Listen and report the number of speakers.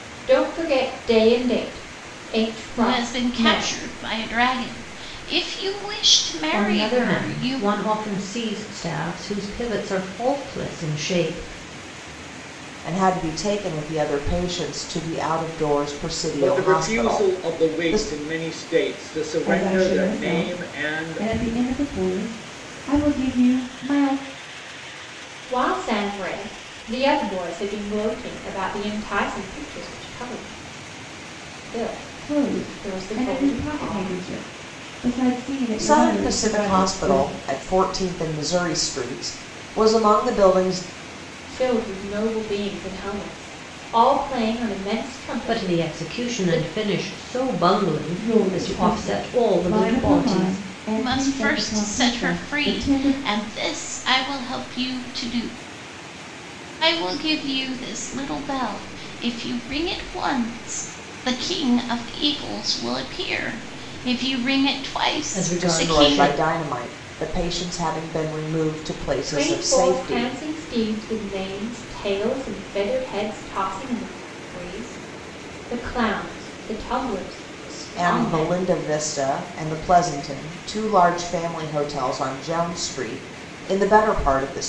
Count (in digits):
6